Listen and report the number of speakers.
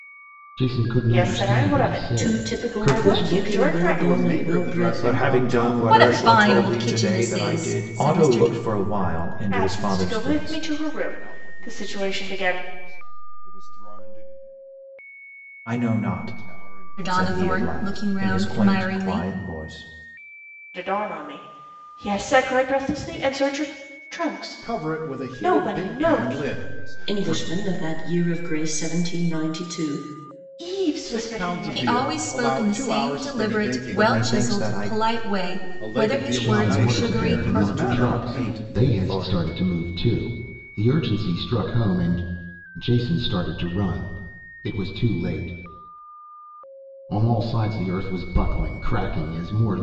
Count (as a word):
seven